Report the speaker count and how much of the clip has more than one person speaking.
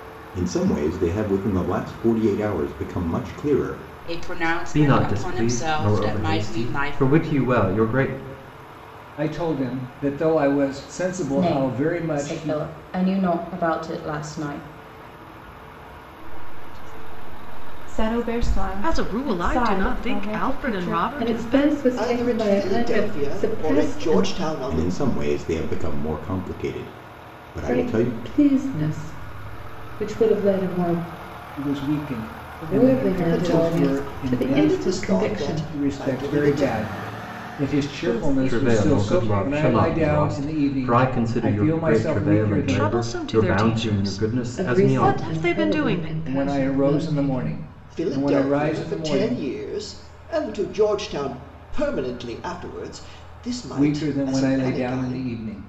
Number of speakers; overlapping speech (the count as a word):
ten, about 52%